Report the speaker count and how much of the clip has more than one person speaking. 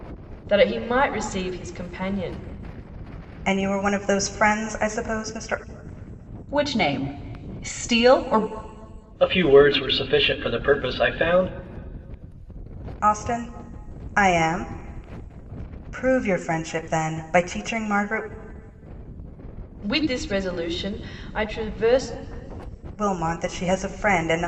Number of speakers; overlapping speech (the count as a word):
four, no overlap